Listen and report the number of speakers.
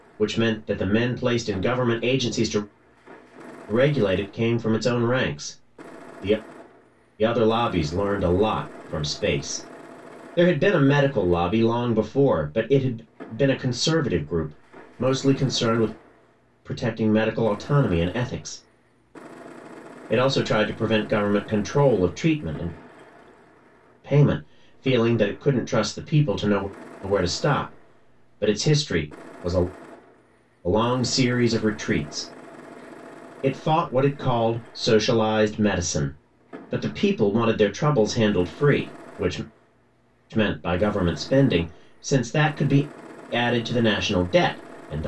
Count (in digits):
1